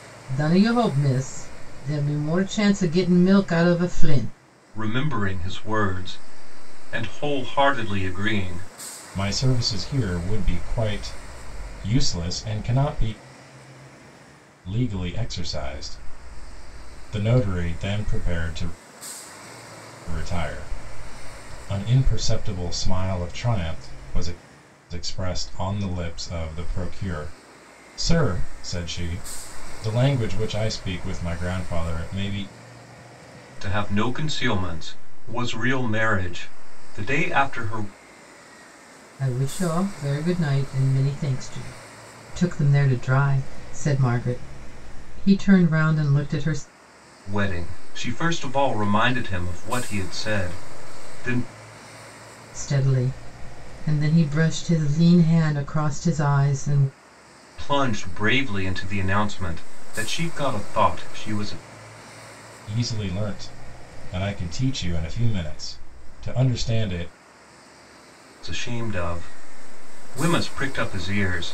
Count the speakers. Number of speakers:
3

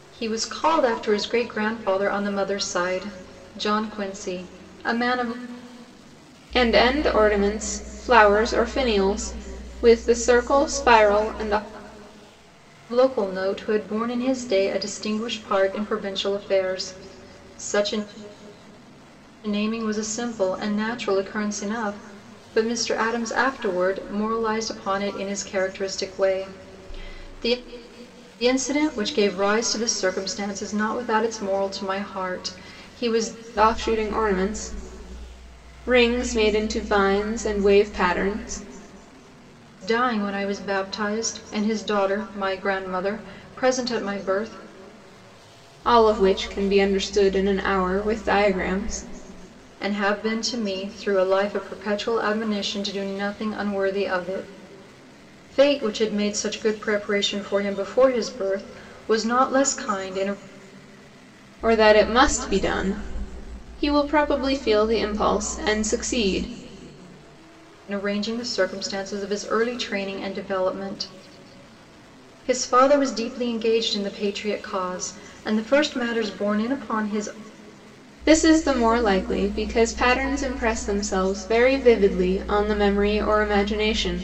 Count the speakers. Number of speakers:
2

